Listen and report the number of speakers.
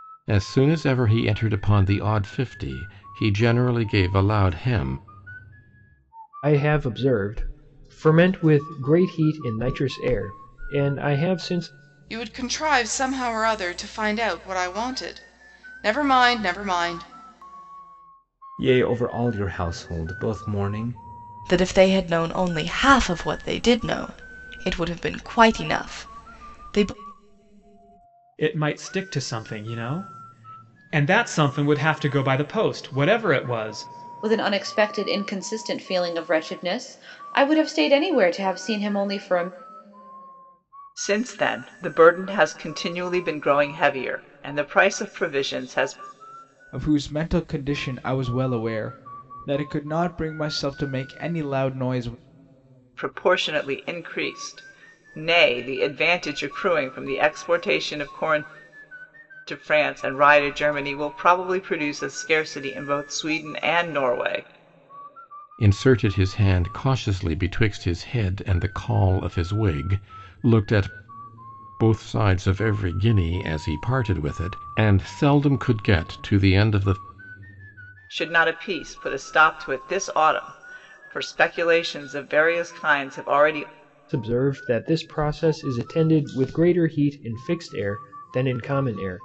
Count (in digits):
9